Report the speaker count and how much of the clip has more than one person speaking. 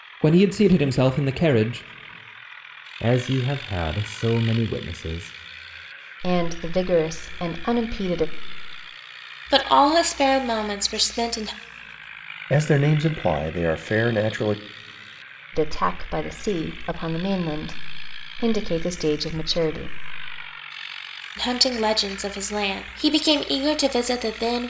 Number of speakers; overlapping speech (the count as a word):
five, no overlap